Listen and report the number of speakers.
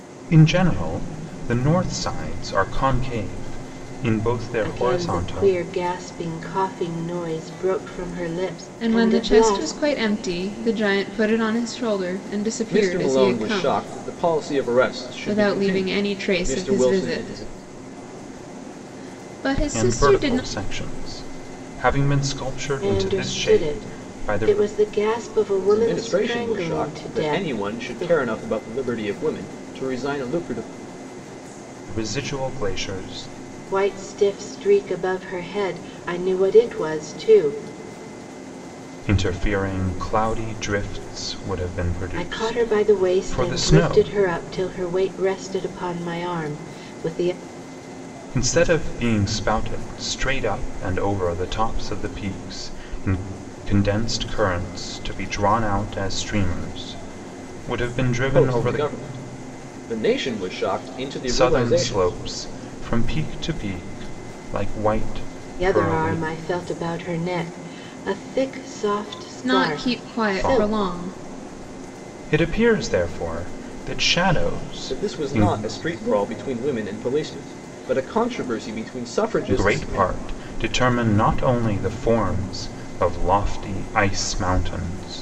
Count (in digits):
4